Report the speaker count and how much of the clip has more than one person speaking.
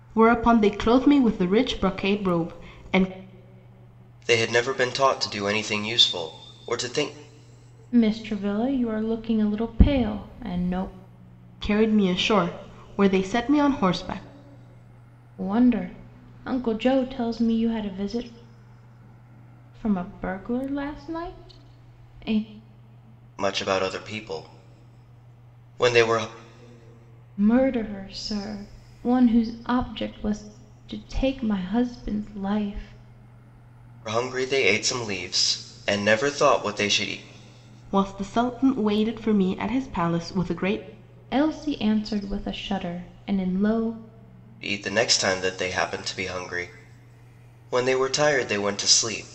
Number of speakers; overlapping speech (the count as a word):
three, no overlap